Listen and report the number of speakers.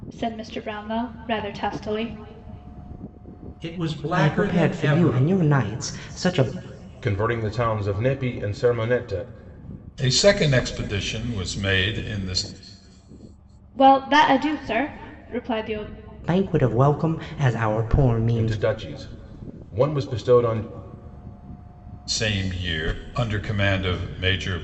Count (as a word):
five